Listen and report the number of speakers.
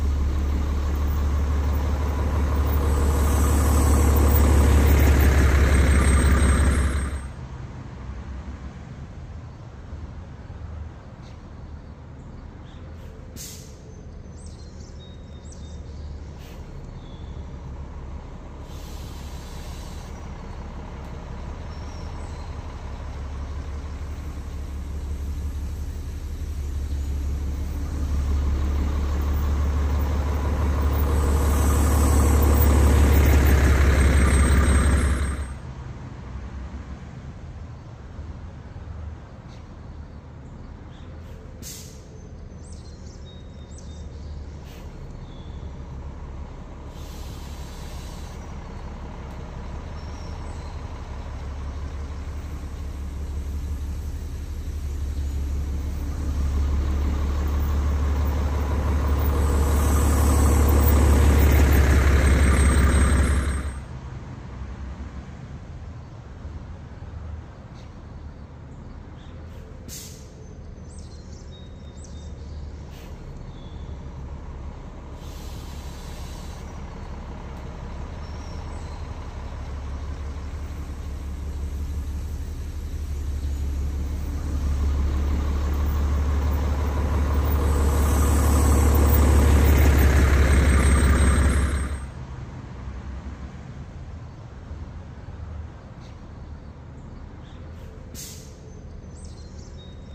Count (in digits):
0